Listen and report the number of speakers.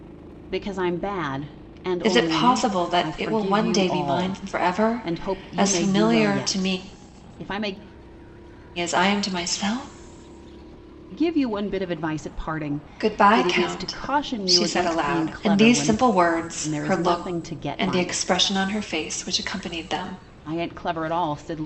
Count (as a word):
two